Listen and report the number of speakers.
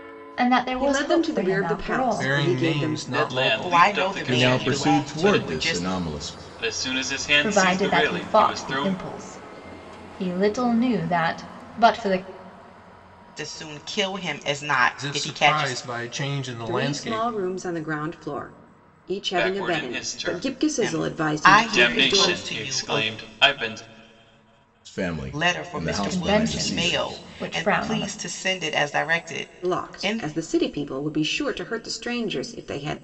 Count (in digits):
6